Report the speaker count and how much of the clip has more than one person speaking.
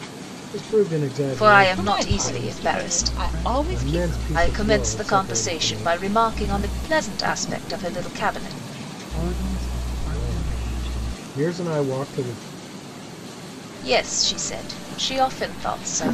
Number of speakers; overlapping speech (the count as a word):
four, about 39%